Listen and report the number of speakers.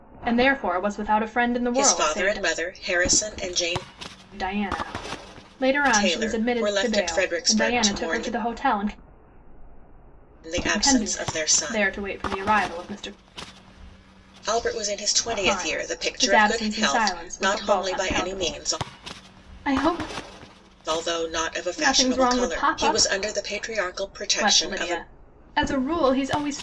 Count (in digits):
2